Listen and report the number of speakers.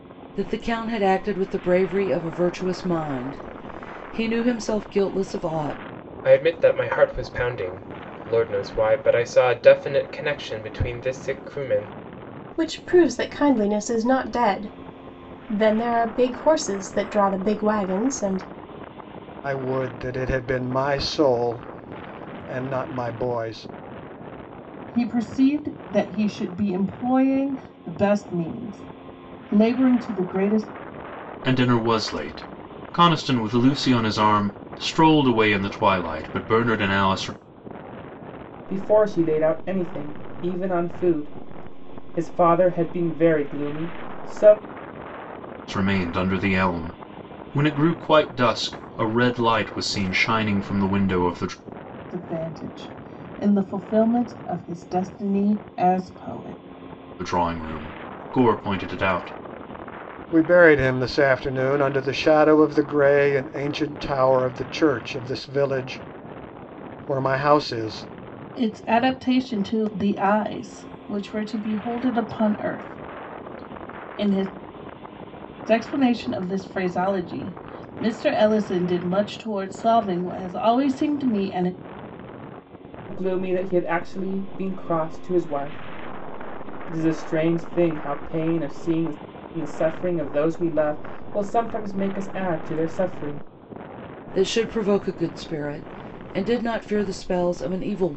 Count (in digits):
7